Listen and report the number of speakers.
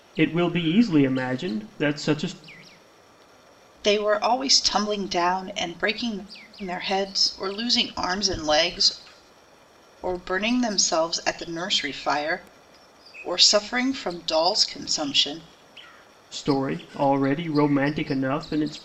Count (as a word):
two